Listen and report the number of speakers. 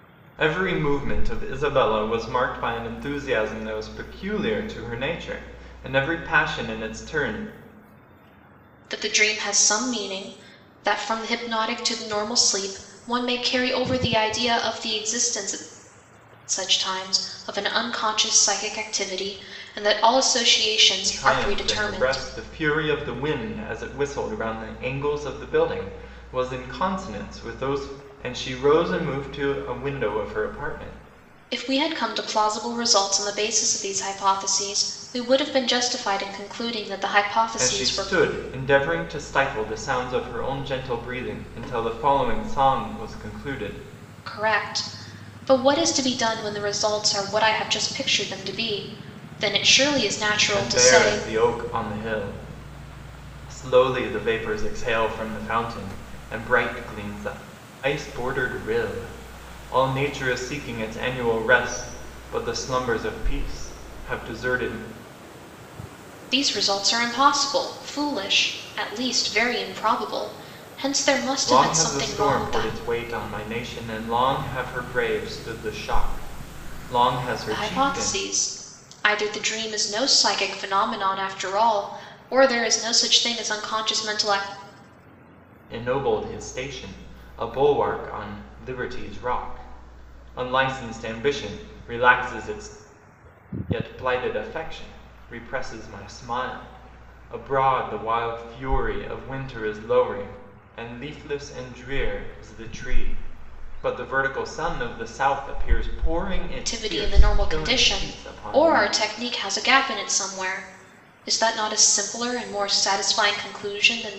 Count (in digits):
2